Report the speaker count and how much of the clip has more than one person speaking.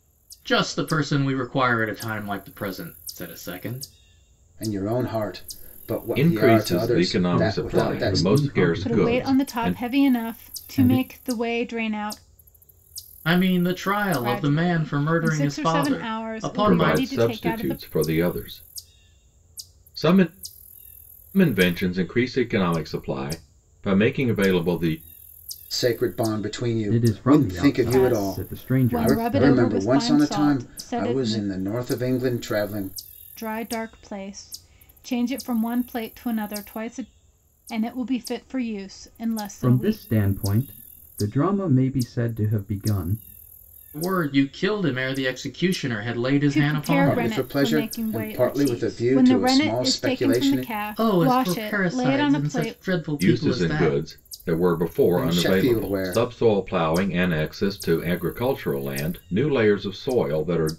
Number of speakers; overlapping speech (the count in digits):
5, about 36%